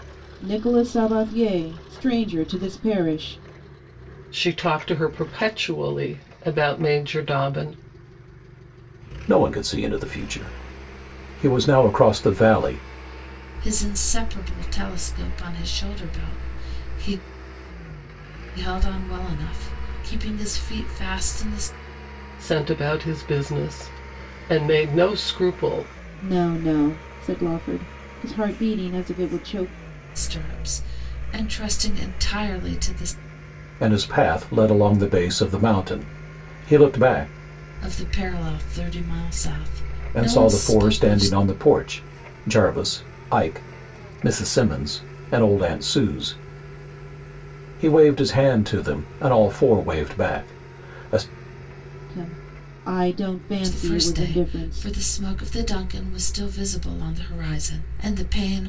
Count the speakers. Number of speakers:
4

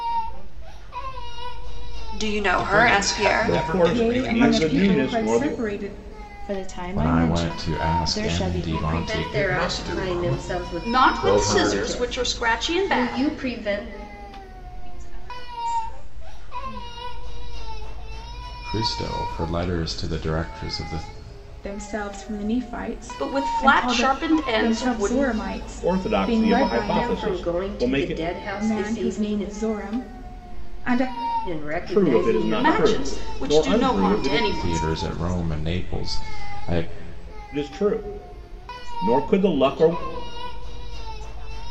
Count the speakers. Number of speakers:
10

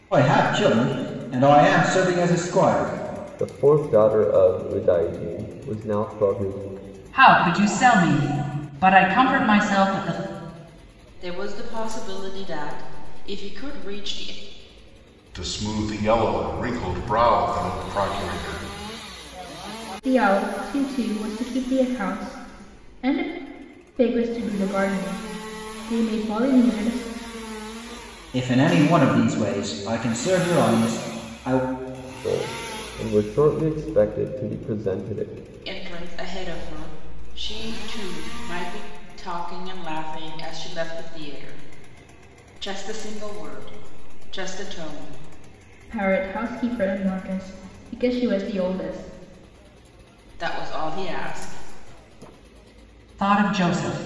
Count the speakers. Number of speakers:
6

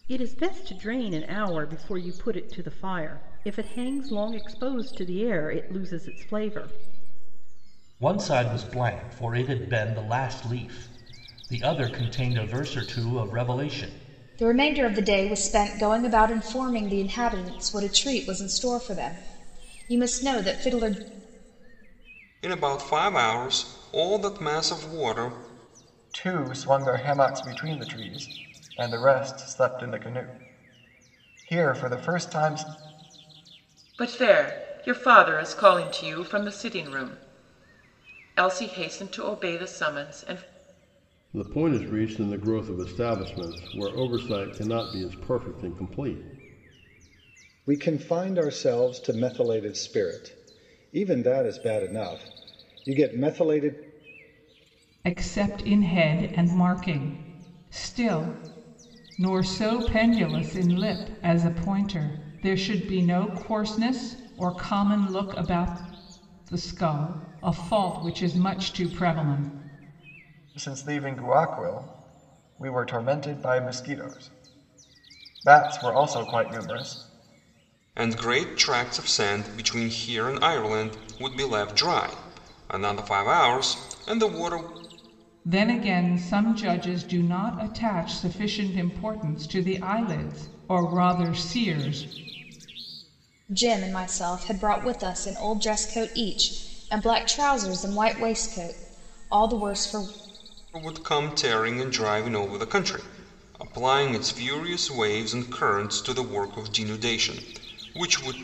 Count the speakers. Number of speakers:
9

